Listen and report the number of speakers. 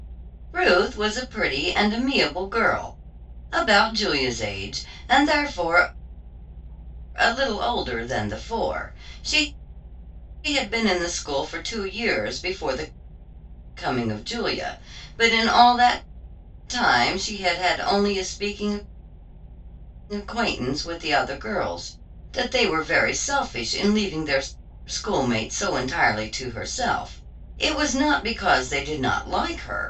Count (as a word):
one